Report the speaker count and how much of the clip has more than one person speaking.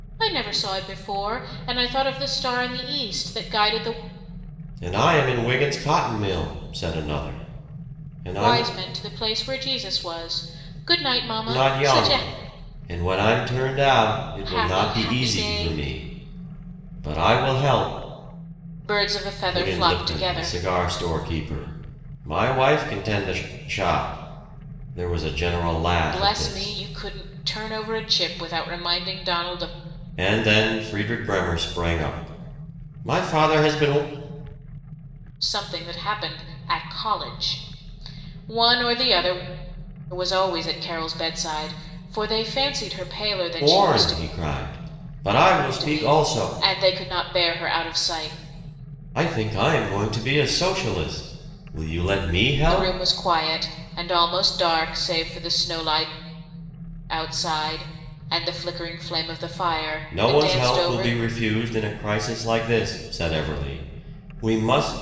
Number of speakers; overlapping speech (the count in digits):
2, about 11%